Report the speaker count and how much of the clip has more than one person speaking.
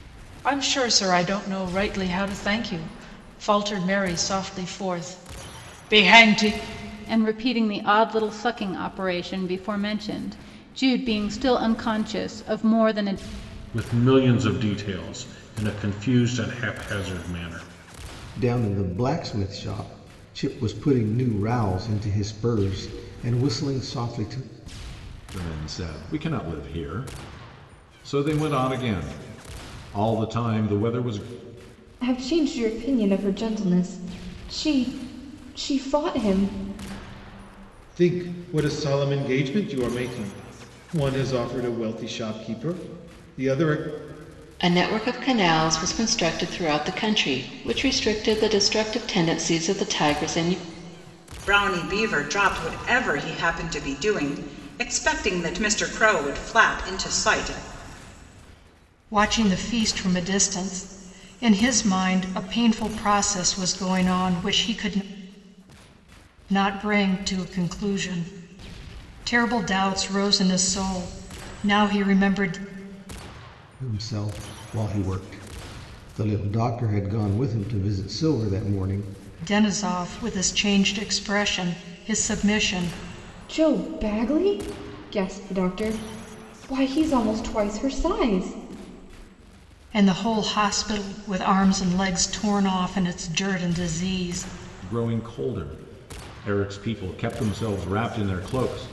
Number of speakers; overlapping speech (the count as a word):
ten, no overlap